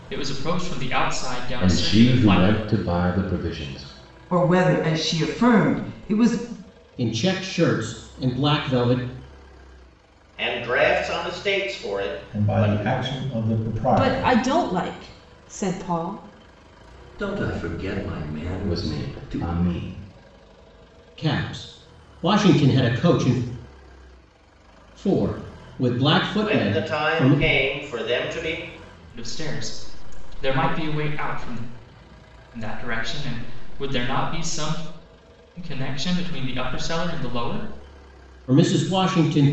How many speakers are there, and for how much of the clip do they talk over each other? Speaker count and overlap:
eight, about 10%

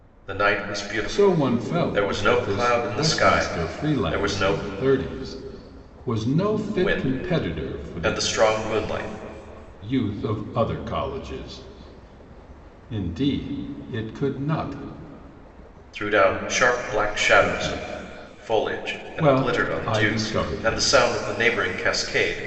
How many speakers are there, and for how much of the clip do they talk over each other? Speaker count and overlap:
two, about 32%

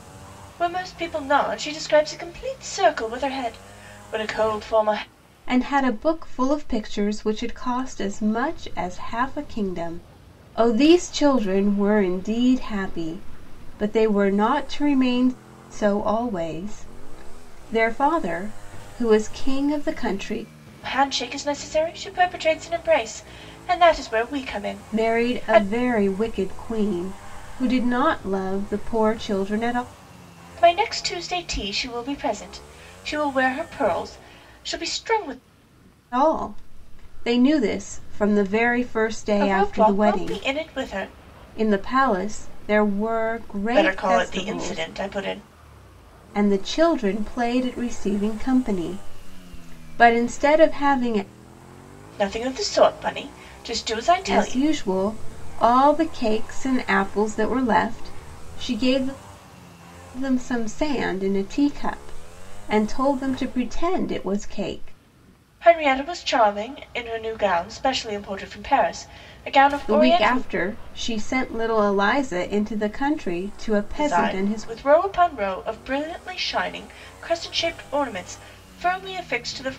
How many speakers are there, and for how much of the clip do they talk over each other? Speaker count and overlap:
two, about 6%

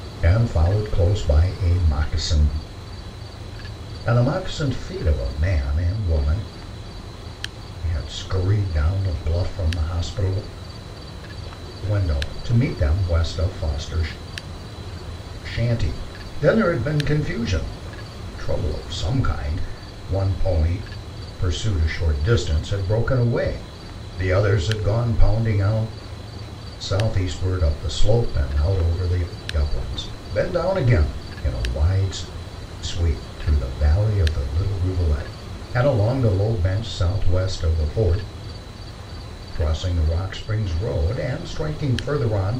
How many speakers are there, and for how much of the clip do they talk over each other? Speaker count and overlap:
one, no overlap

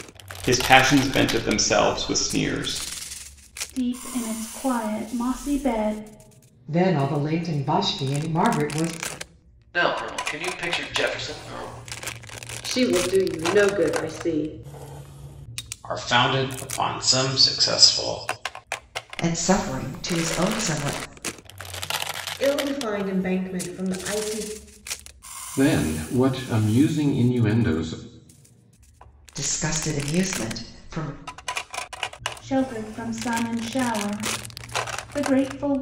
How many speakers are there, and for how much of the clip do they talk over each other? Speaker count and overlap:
nine, no overlap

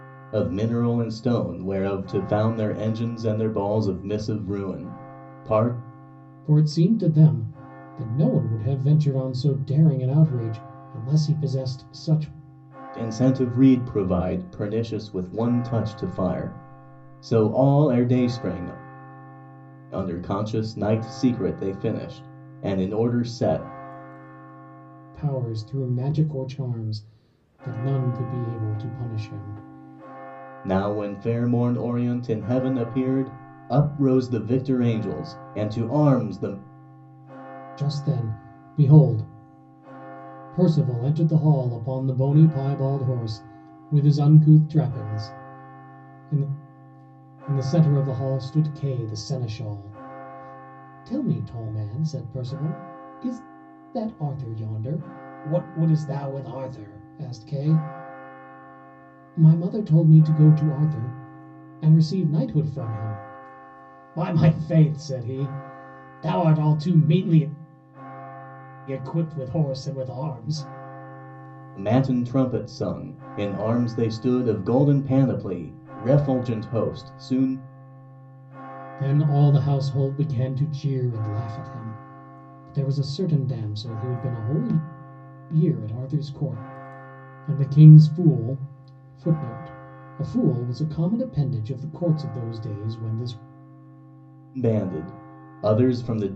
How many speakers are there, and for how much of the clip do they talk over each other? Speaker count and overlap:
two, no overlap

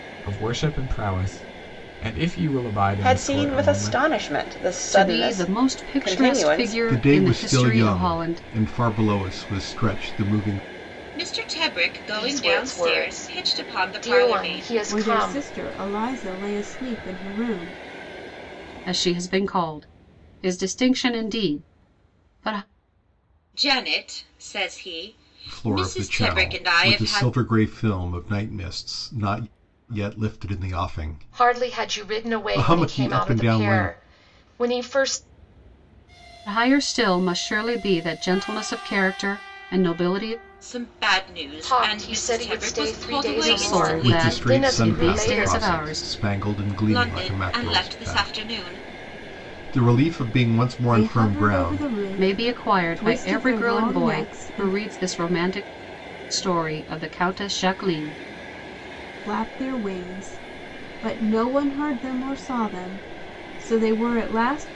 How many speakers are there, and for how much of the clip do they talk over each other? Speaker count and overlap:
seven, about 35%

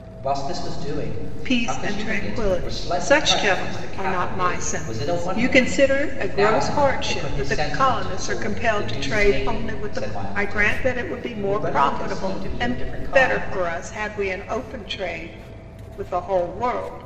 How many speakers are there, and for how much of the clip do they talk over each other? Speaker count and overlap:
two, about 66%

